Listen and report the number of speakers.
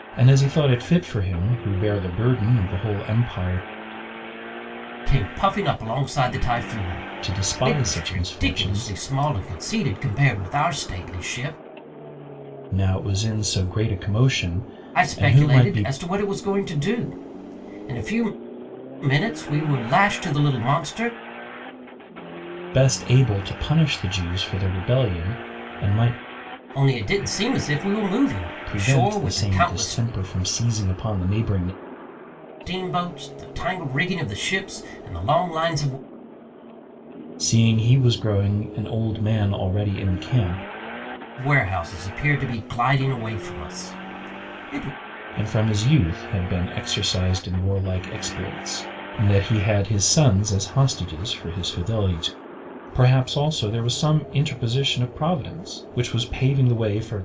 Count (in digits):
2